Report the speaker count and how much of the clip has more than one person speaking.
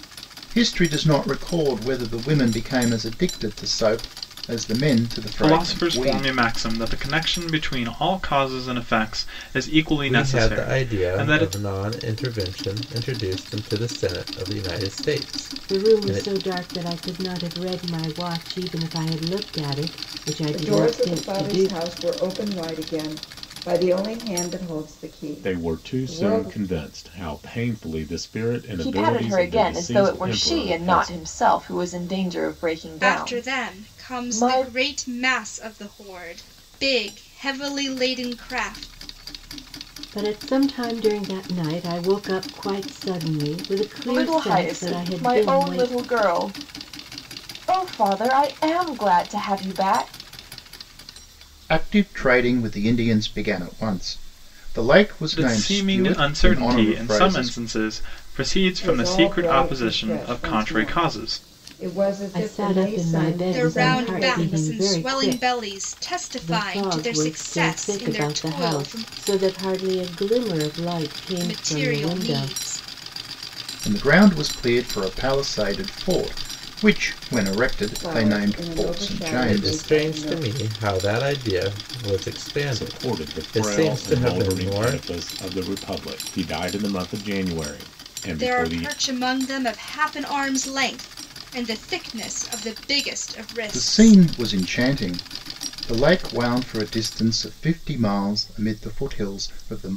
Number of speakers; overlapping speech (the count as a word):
eight, about 30%